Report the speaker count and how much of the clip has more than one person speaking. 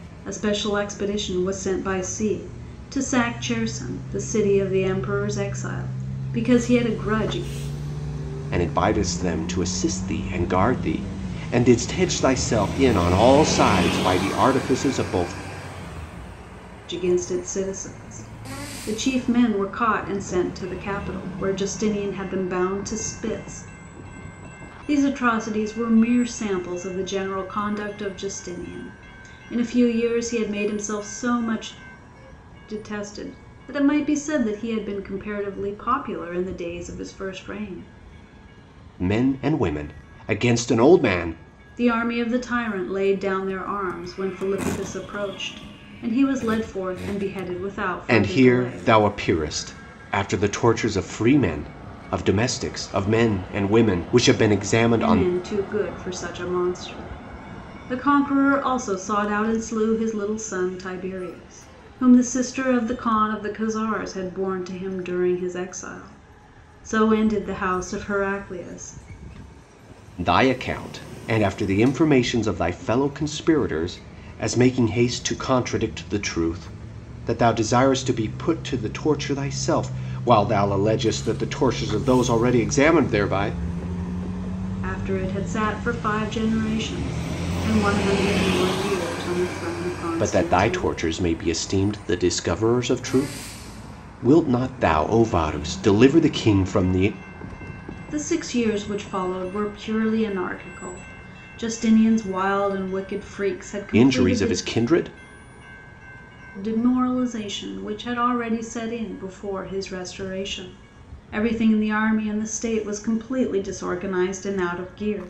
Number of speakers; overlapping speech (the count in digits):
2, about 3%